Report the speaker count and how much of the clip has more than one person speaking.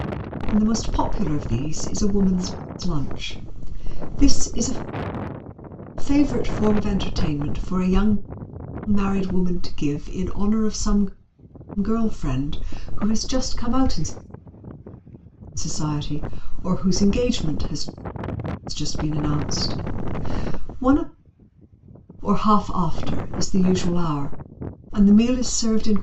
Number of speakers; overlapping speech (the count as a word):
one, no overlap